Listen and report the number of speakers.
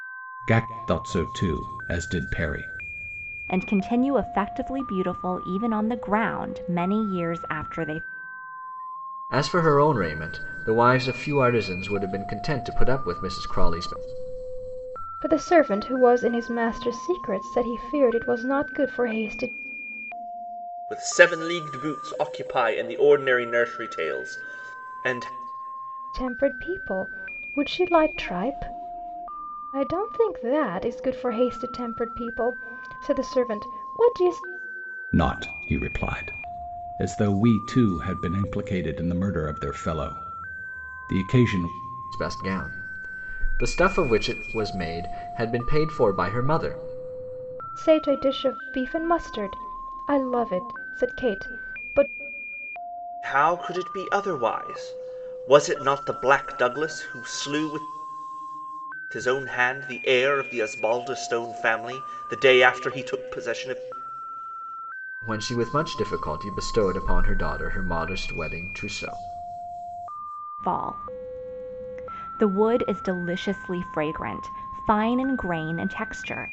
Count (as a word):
five